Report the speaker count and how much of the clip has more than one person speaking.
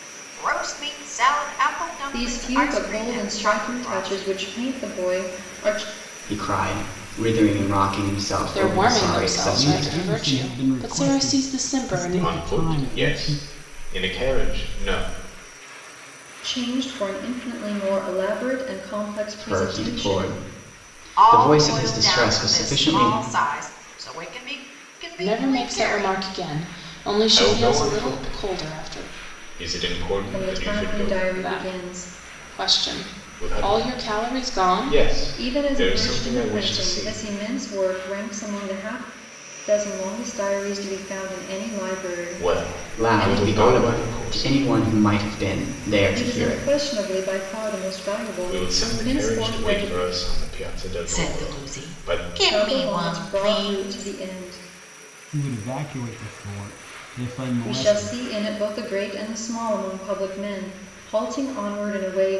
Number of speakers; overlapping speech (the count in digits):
6, about 41%